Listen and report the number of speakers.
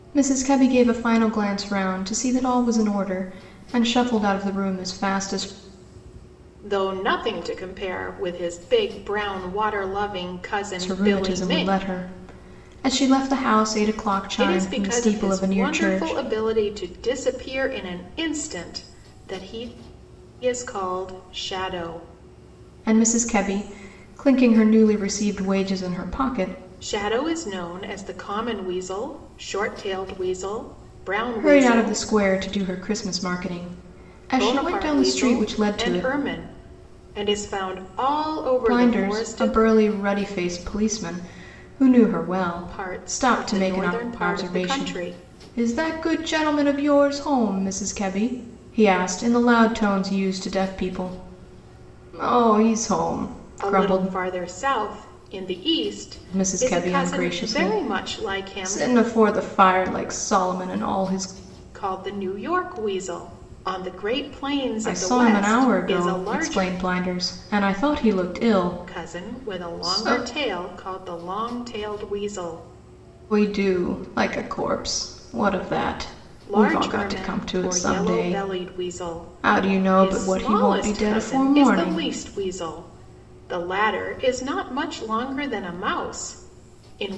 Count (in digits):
2